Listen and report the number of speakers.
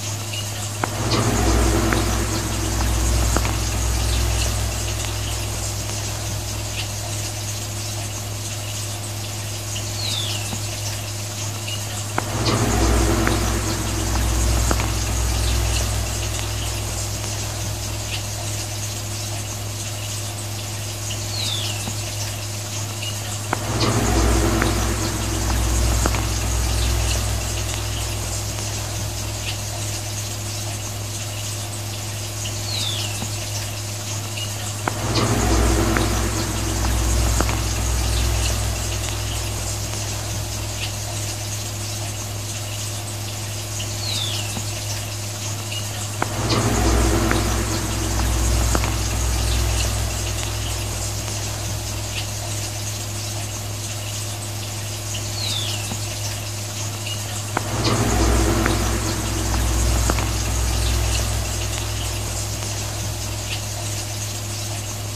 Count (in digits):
0